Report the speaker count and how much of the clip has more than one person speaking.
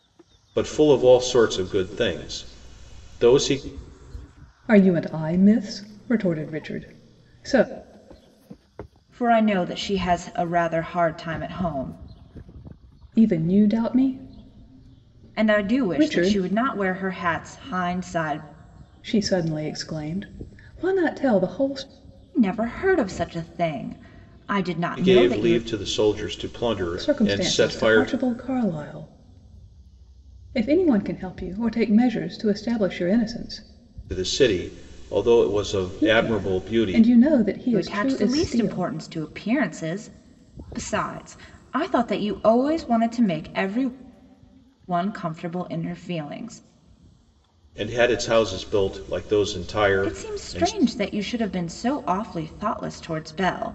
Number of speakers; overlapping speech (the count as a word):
three, about 11%